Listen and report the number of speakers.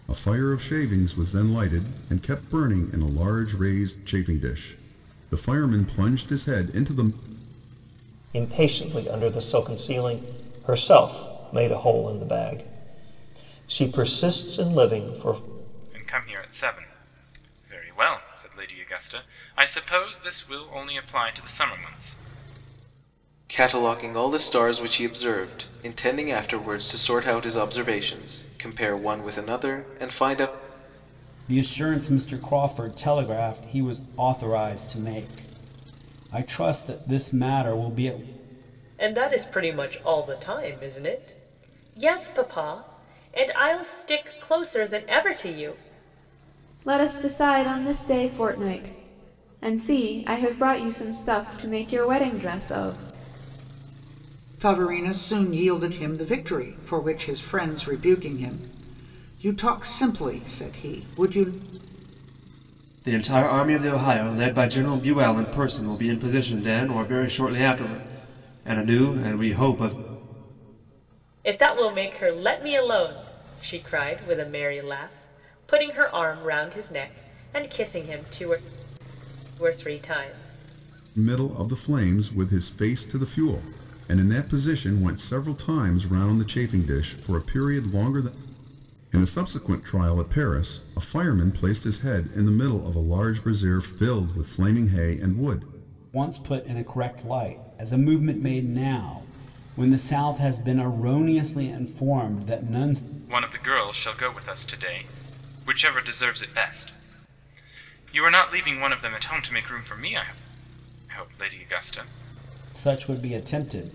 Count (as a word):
nine